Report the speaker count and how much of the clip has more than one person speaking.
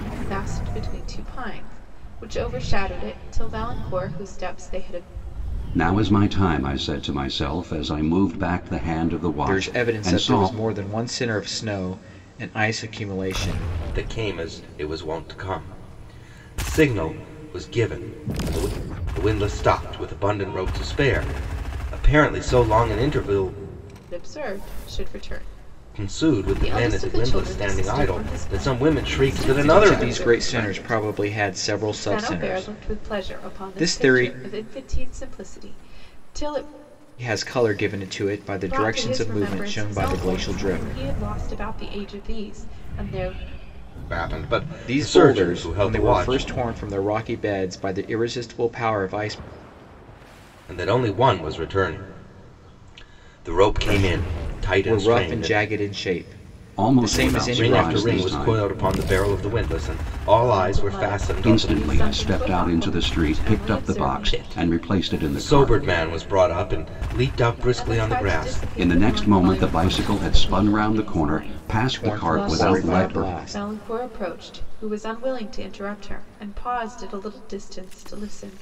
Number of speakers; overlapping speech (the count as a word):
four, about 35%